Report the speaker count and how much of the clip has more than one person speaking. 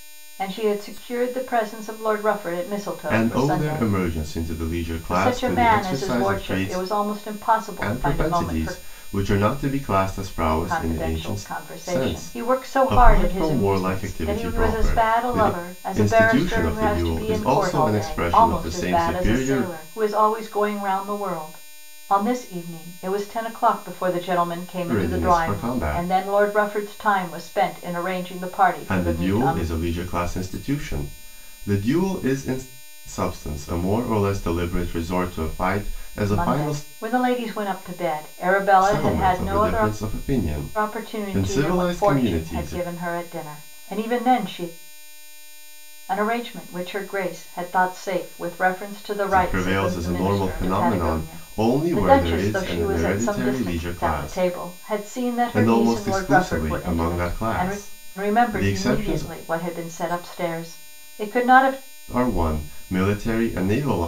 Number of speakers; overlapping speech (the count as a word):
two, about 41%